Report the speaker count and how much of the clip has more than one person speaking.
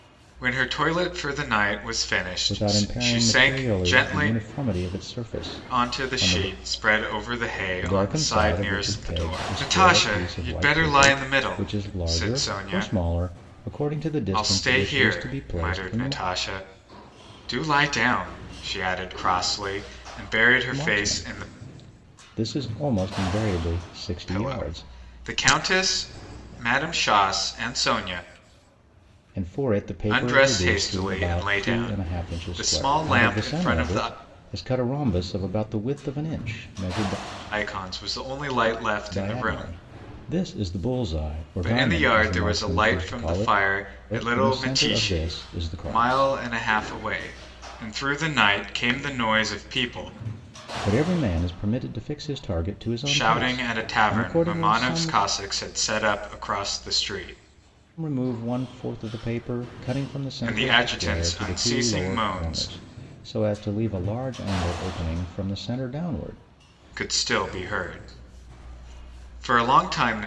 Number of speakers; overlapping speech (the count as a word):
two, about 35%